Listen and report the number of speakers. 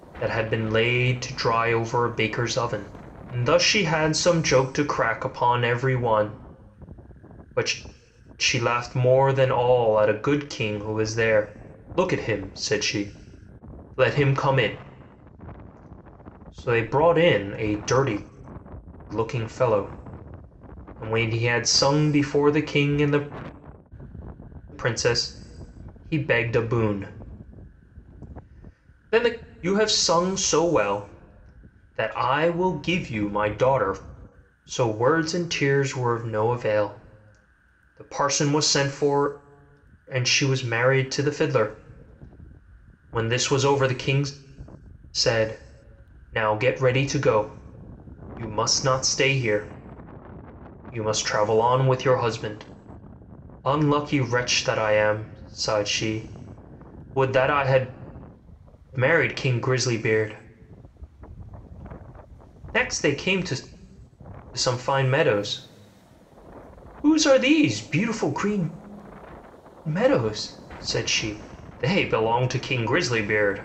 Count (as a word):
one